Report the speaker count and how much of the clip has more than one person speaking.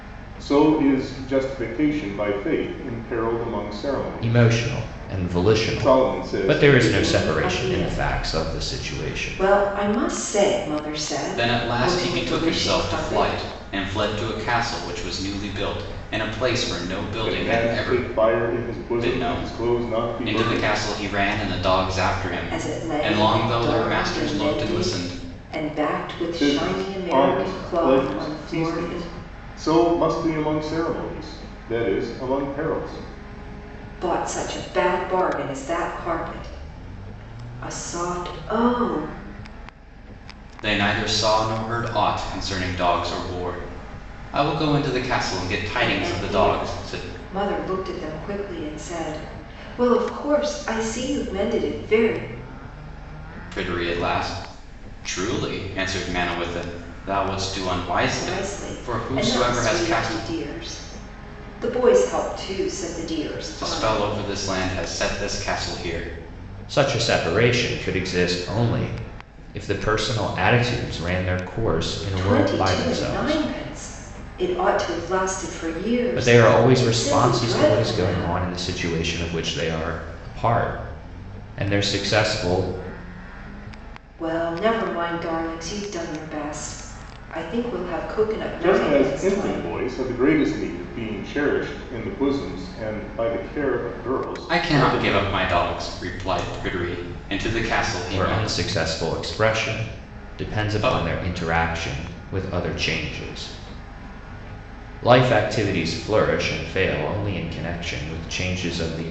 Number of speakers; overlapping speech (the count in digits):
4, about 26%